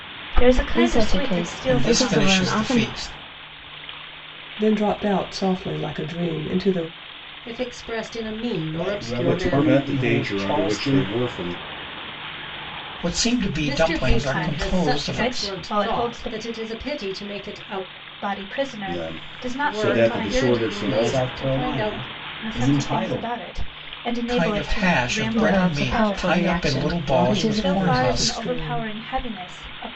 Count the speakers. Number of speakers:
7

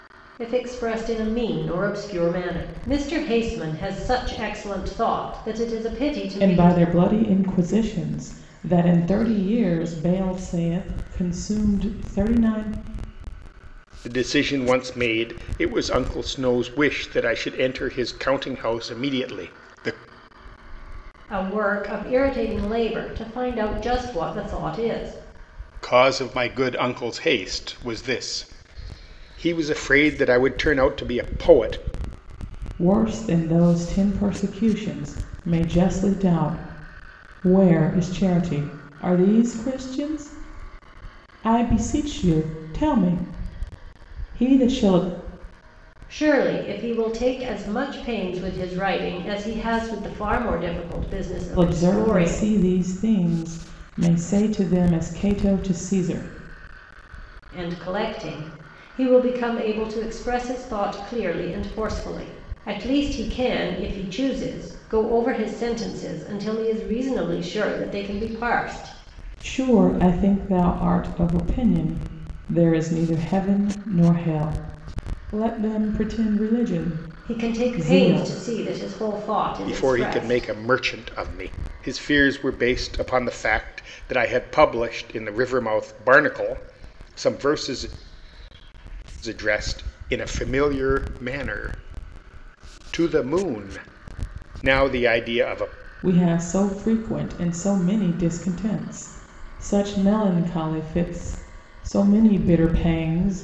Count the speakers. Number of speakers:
3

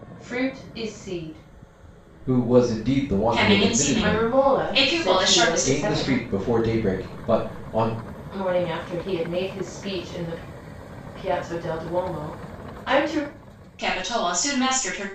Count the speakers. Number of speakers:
3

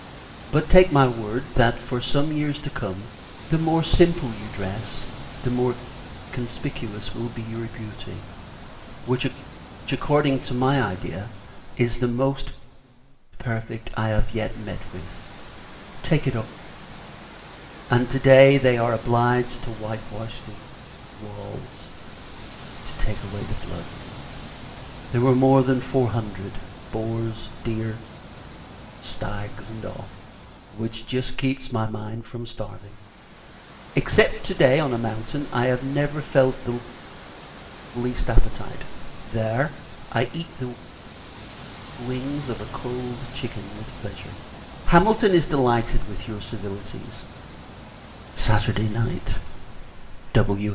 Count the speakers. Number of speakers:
1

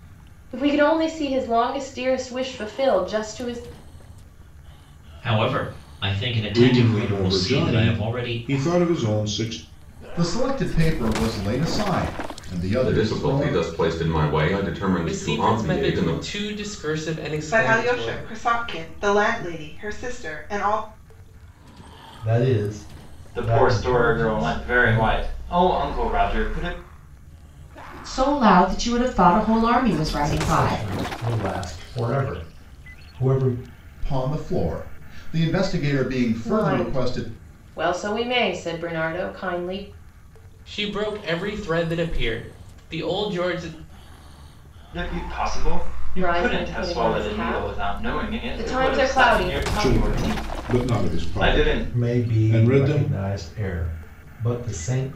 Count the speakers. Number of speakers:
10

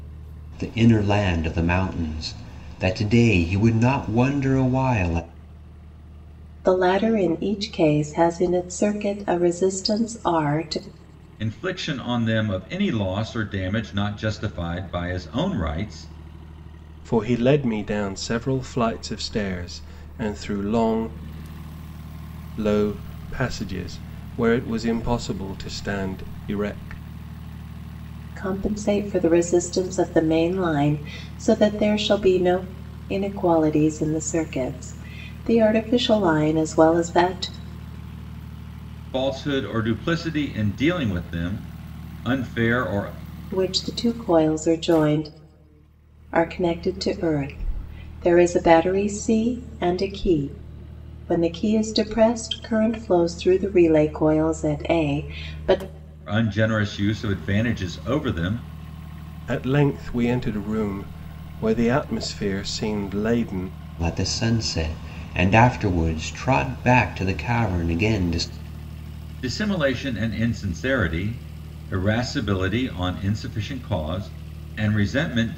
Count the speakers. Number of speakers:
4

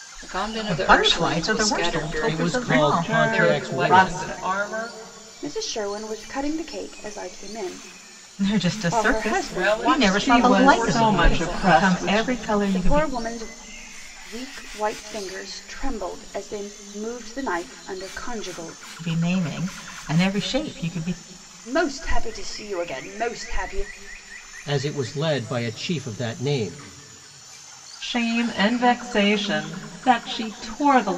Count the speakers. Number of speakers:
6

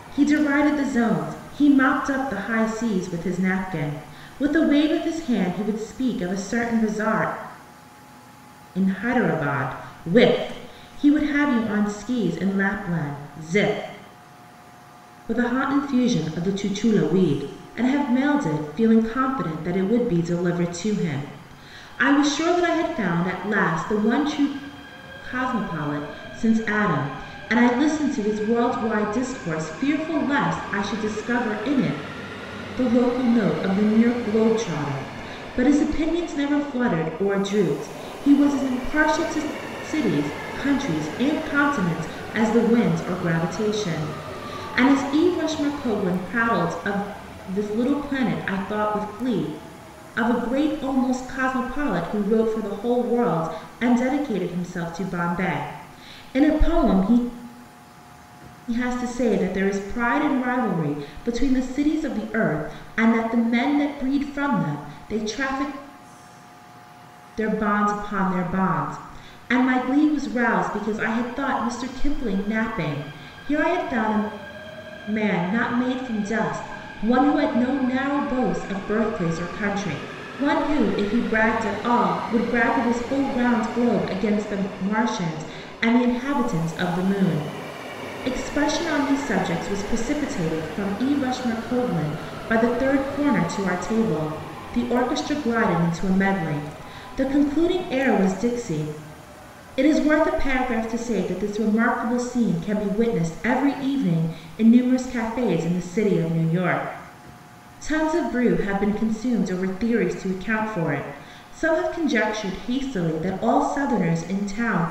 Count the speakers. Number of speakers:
1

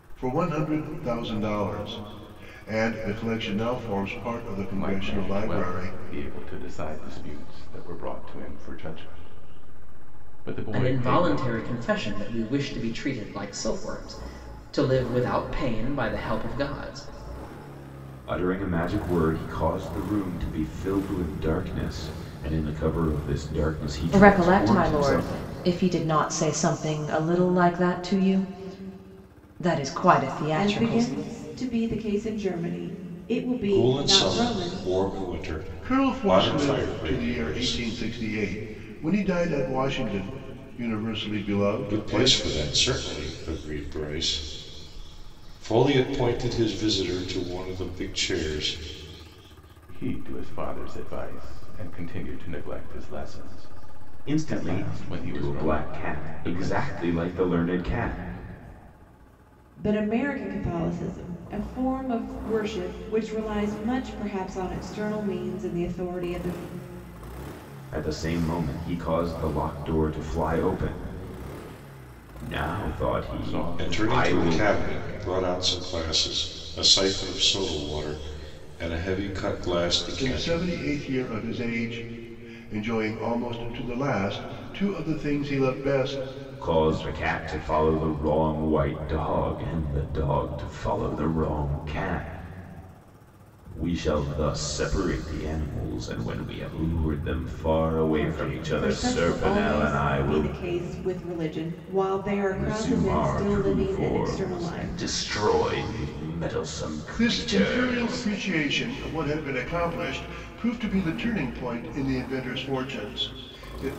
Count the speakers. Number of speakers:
7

